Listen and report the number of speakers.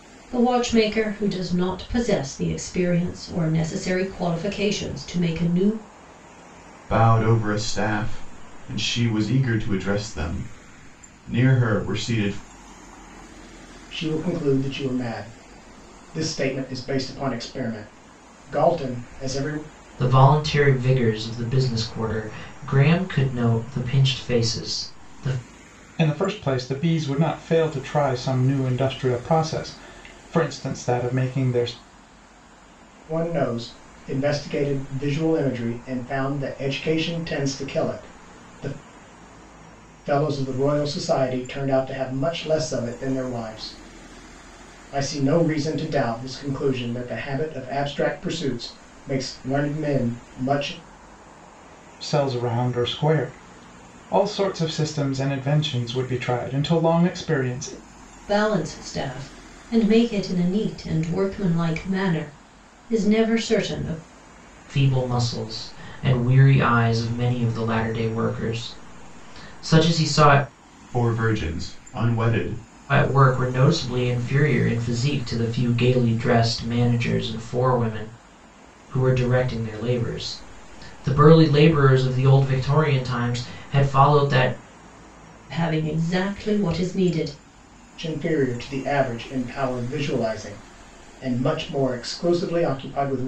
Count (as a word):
five